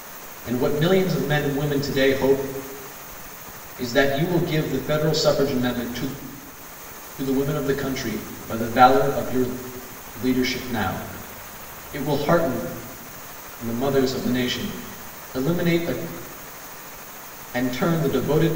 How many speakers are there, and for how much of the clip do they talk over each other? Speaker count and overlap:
one, no overlap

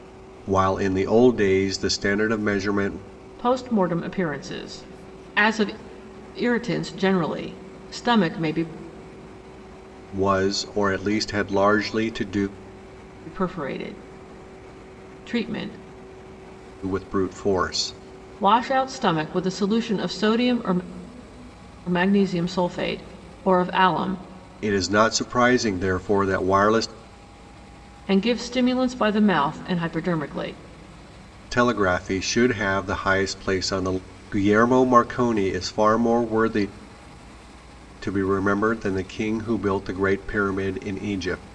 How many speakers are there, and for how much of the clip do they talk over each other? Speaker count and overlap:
two, no overlap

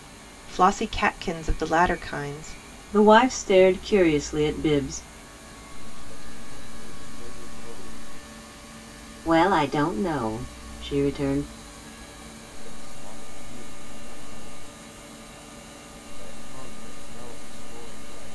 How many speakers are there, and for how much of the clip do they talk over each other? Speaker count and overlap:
three, no overlap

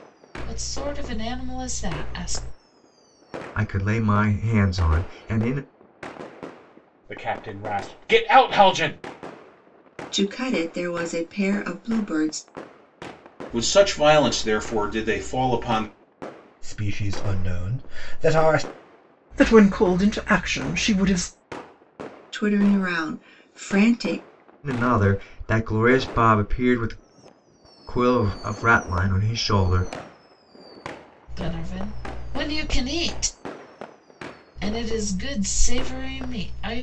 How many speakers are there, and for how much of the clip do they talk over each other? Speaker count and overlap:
seven, no overlap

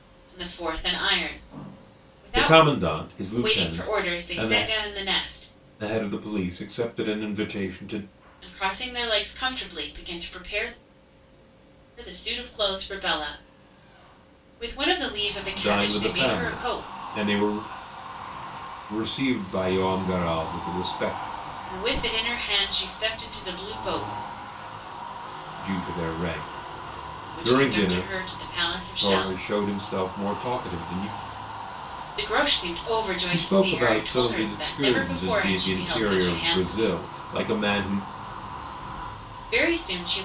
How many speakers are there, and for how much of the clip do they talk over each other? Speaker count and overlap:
two, about 20%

